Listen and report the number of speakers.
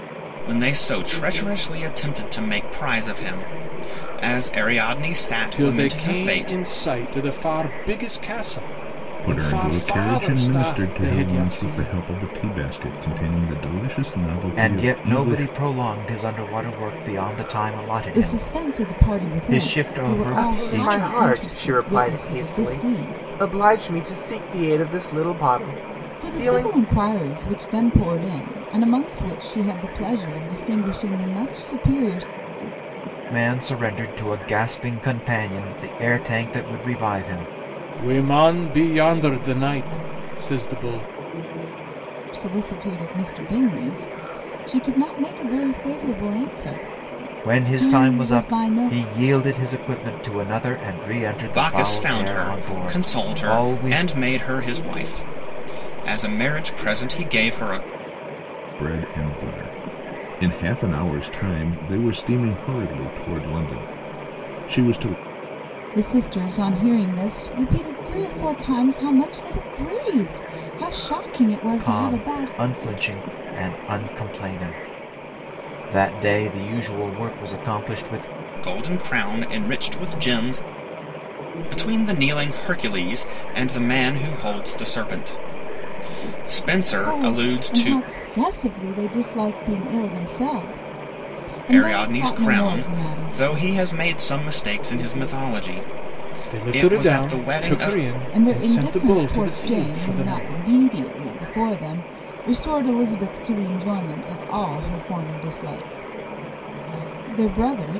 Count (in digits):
6